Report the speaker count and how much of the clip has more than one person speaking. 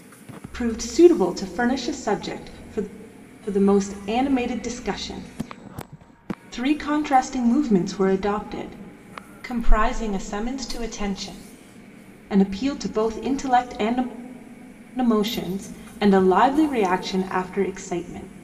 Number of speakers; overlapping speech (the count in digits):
1, no overlap